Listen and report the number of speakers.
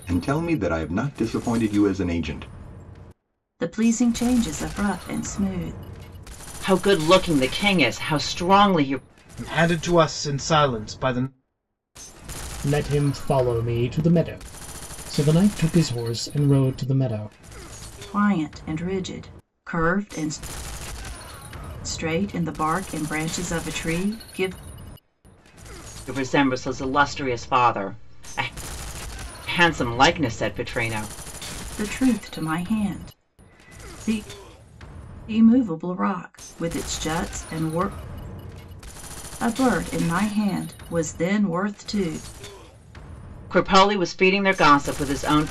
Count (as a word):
five